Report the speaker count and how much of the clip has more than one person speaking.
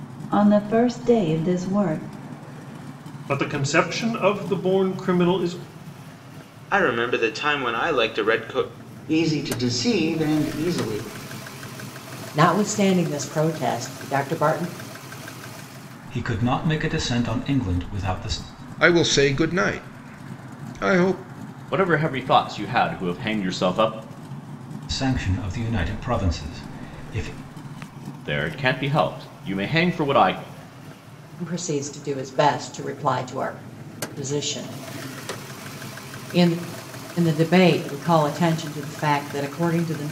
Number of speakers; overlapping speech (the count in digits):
8, no overlap